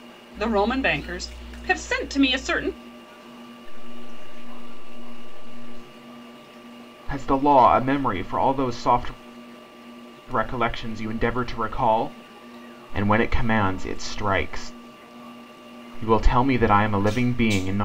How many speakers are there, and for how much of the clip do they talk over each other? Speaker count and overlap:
three, no overlap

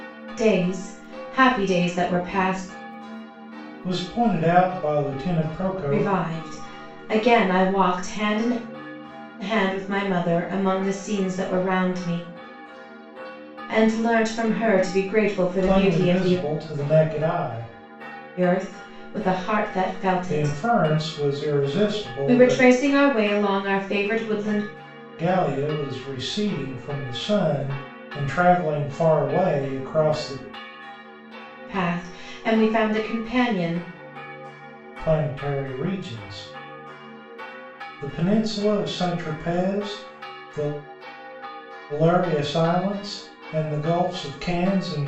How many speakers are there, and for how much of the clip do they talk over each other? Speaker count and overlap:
two, about 5%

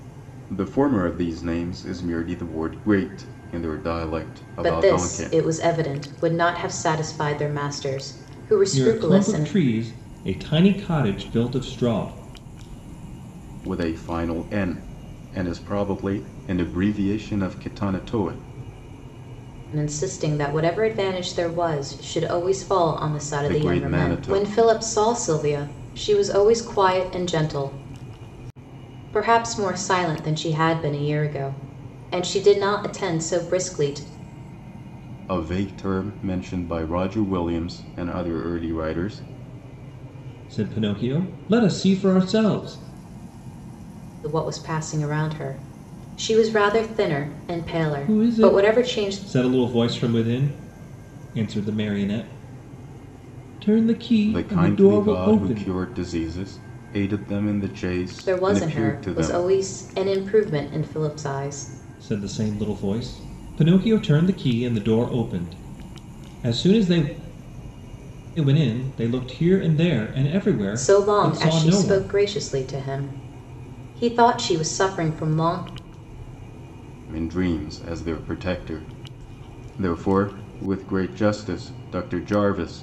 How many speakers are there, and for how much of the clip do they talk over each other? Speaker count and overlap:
three, about 10%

